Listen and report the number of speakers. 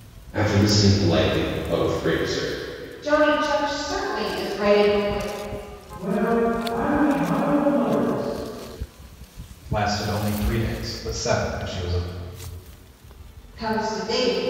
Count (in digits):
4